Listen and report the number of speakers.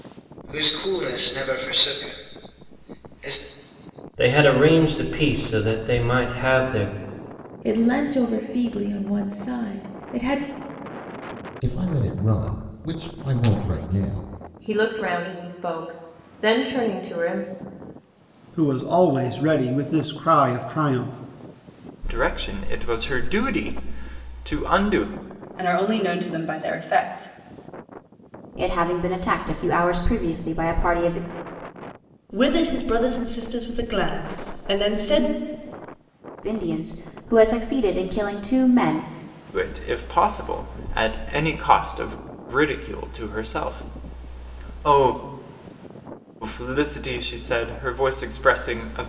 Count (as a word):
ten